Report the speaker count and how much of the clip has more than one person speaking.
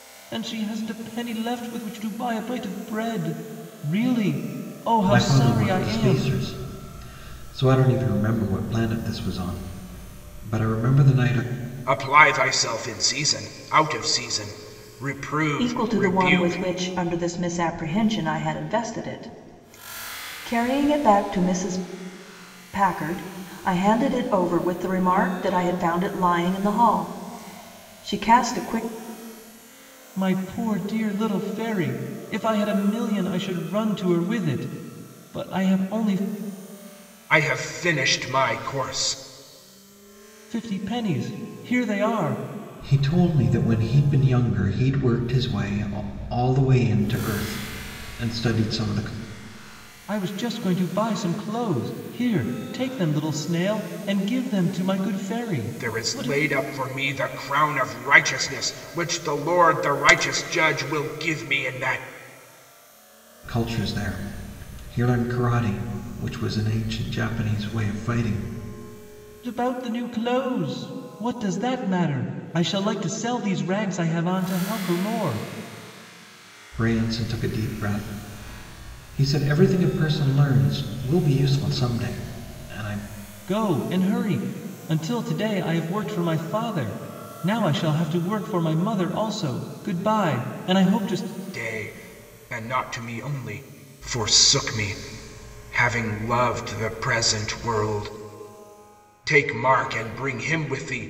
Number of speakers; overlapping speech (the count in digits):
4, about 3%